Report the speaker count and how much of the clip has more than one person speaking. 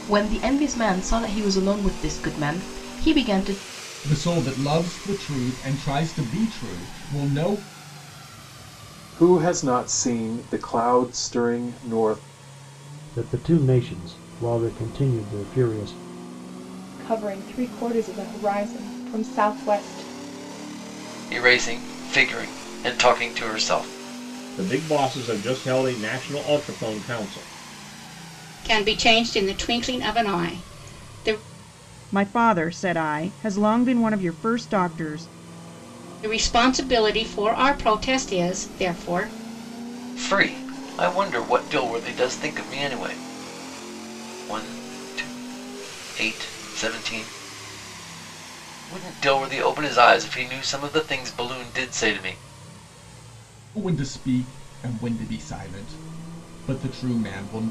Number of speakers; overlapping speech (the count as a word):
nine, no overlap